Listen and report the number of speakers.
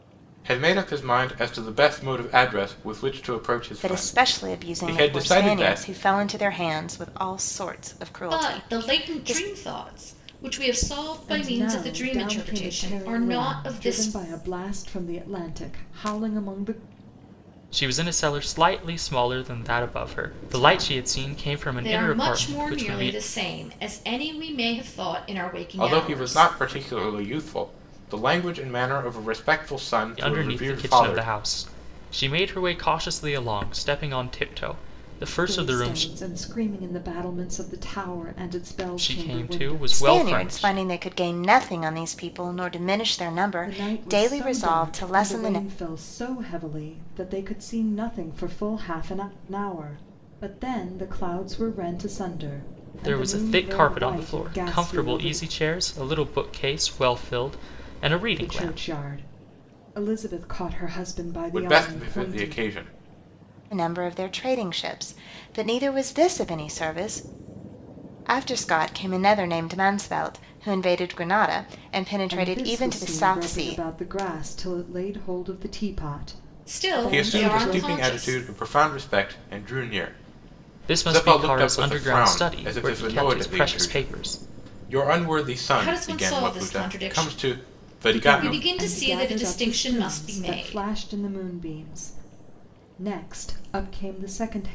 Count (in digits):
5